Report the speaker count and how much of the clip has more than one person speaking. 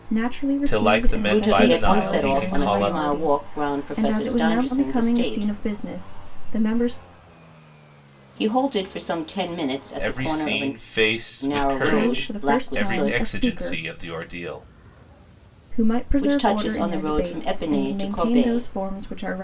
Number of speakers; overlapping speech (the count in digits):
3, about 55%